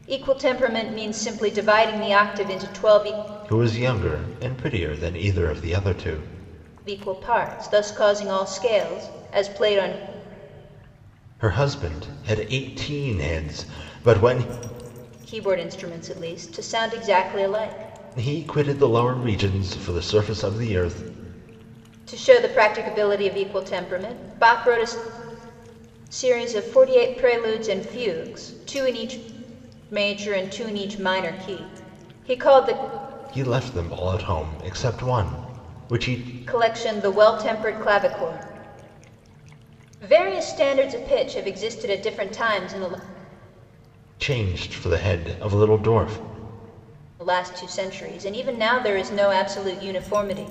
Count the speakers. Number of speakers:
two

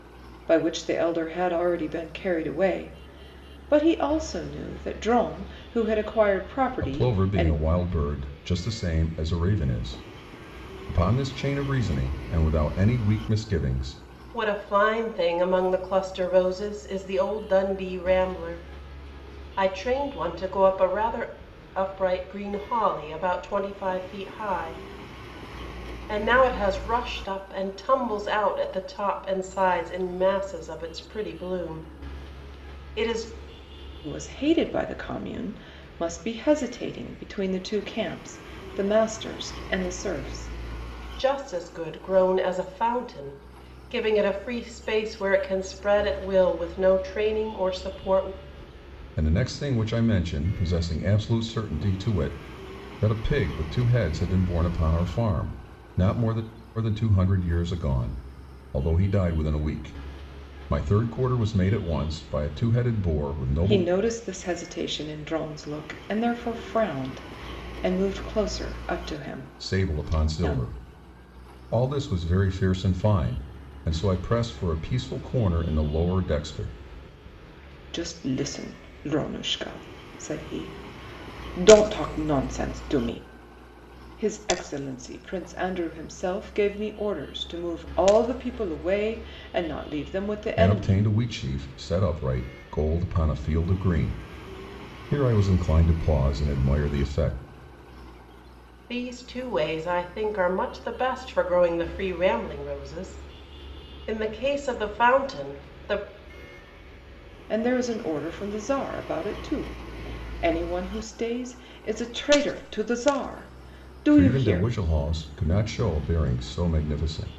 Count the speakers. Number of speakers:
three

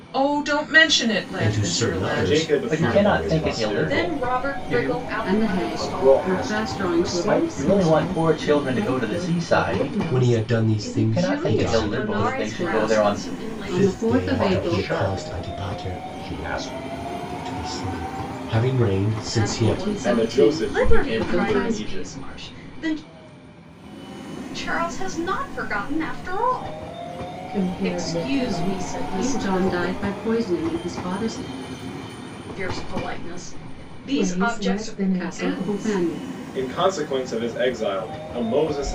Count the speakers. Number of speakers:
eight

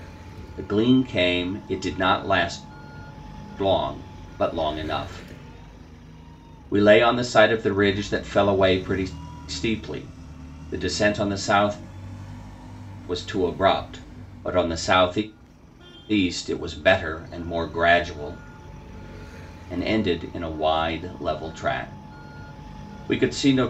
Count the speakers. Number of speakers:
one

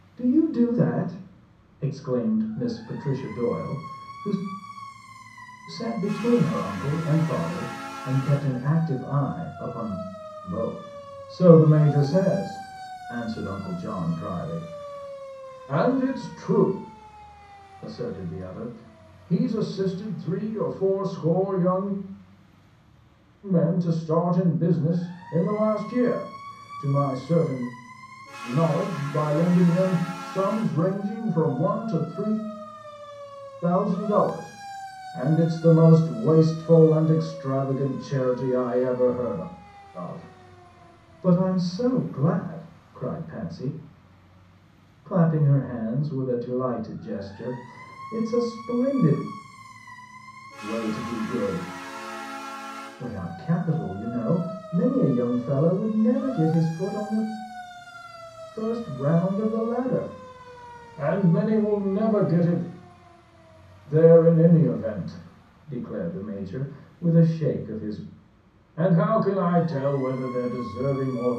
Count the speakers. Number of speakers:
one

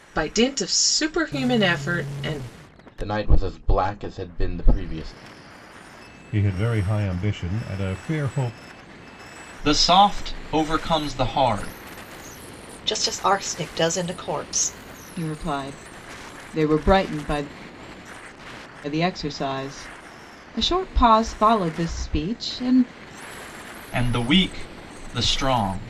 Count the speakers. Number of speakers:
six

